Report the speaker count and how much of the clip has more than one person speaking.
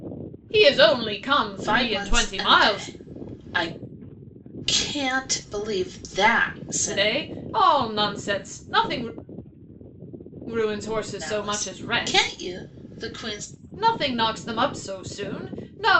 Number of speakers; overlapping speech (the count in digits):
2, about 18%